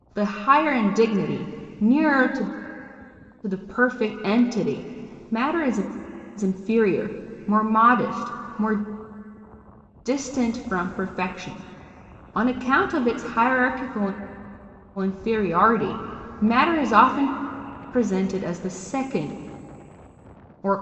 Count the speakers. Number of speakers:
1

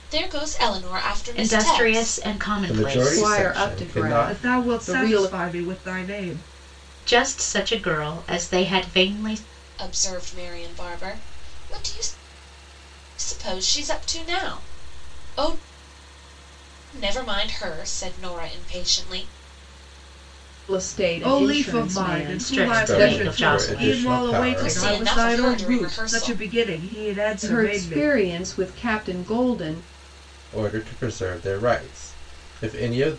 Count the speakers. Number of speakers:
5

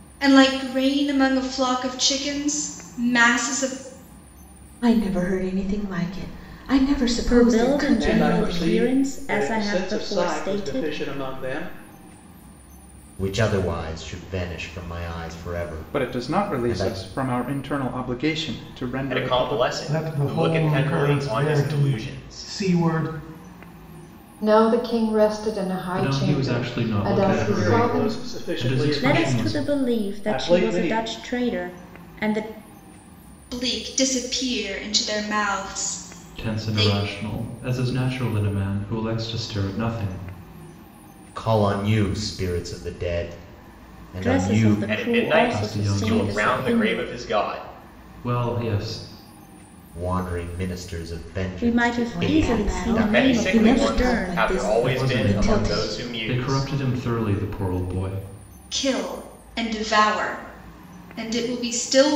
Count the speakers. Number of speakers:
10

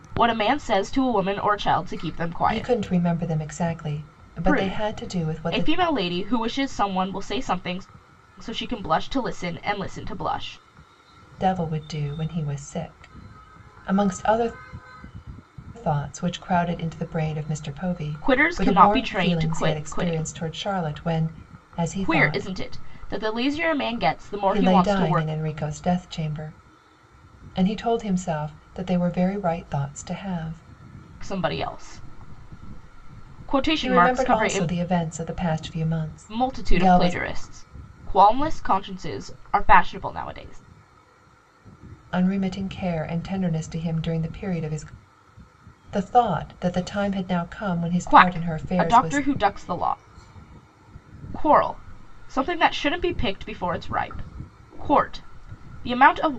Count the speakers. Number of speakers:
2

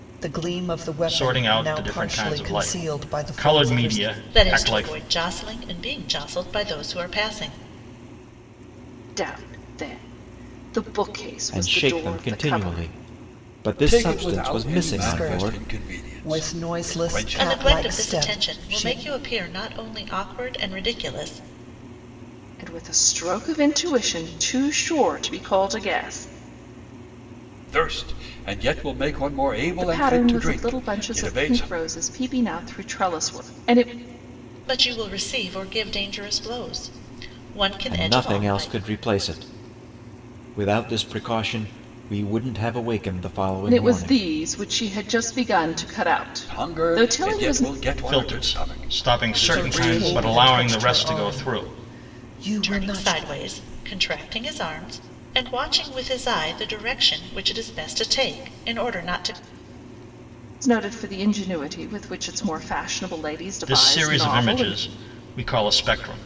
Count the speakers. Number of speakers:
6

